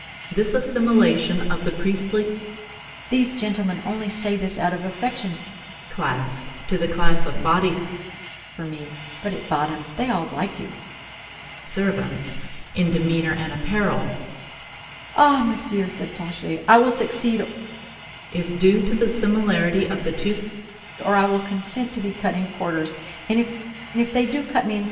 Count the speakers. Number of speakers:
2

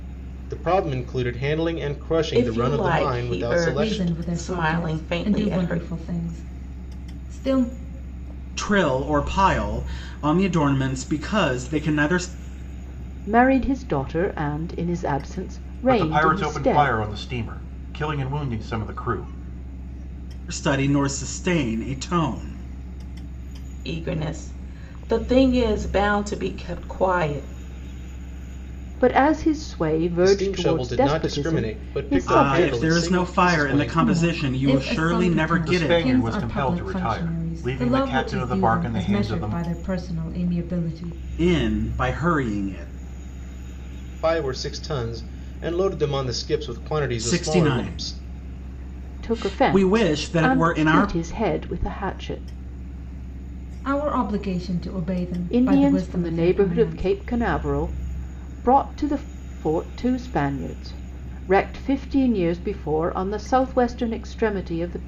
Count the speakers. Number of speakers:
6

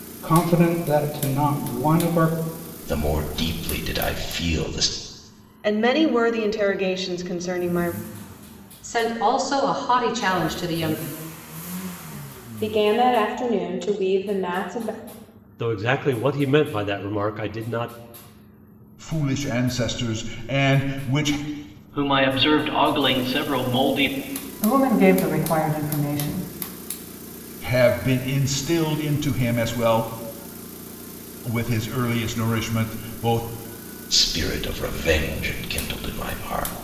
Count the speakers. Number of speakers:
9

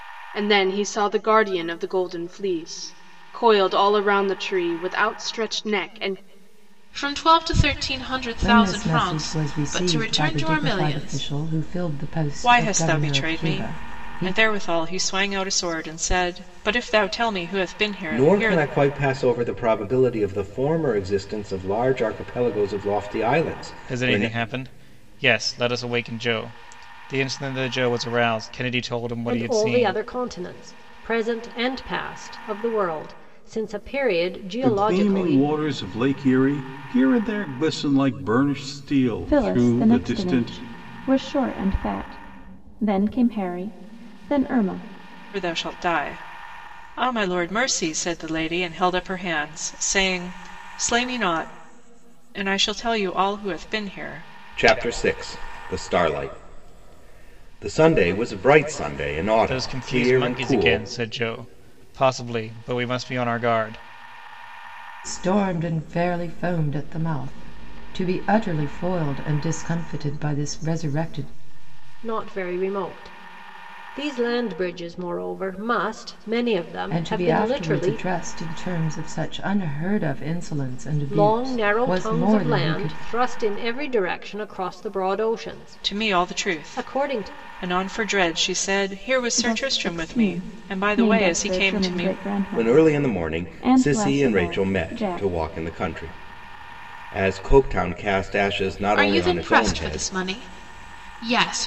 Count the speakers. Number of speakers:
9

